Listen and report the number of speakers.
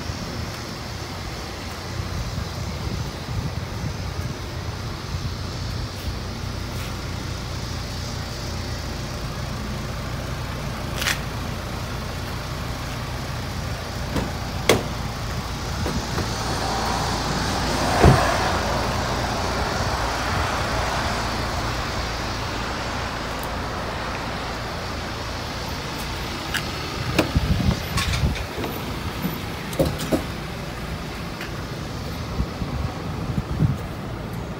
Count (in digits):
0